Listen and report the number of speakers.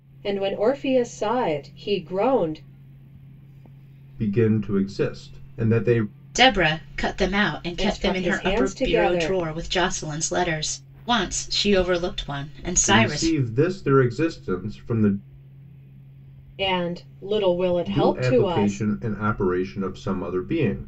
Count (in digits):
3